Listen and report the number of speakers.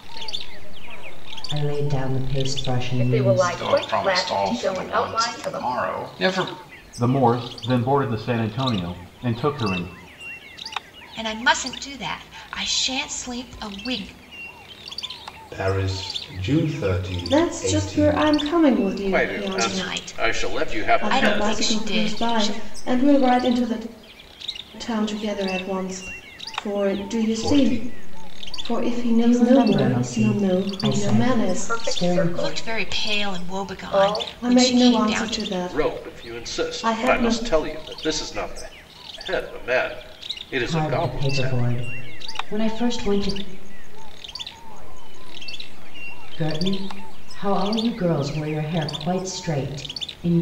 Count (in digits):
9